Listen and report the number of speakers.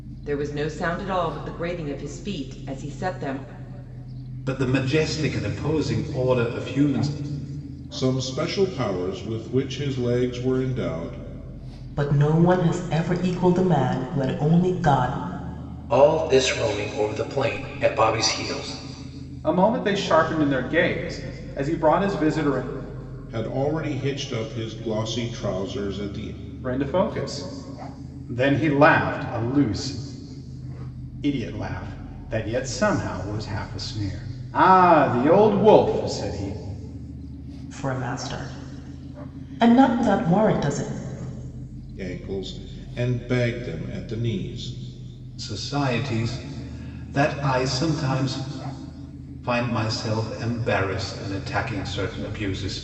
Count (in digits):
6